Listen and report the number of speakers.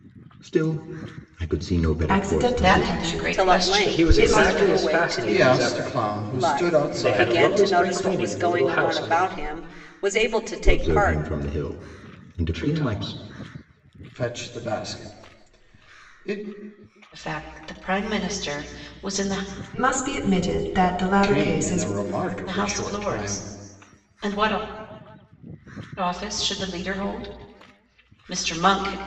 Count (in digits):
6